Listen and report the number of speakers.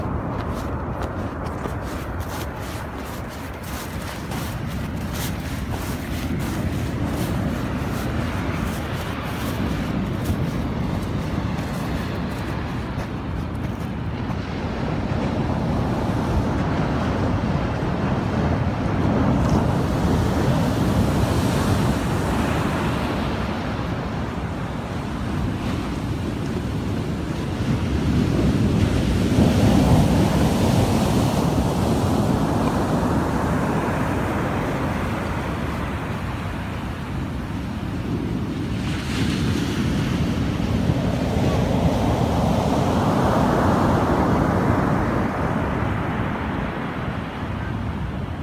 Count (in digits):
0